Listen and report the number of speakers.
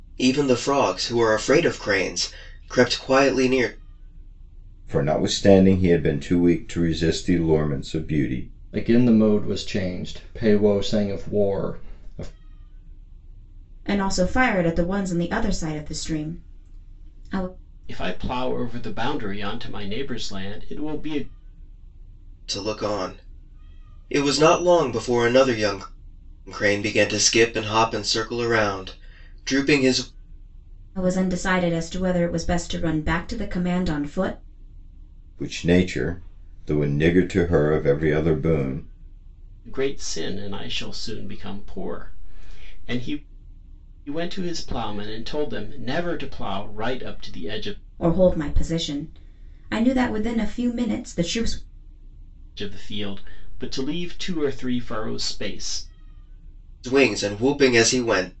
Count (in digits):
5